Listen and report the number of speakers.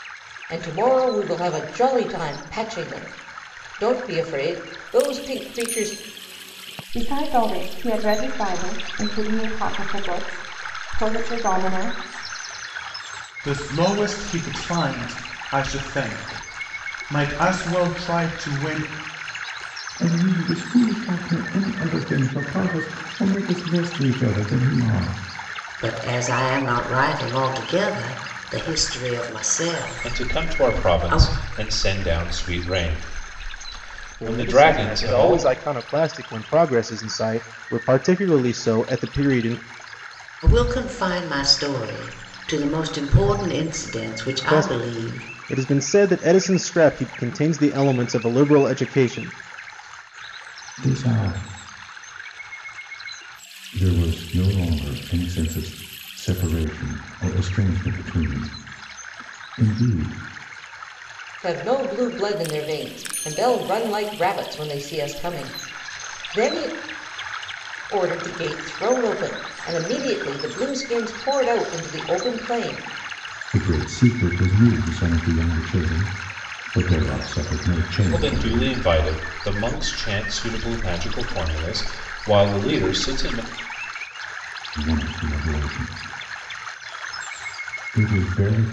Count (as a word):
seven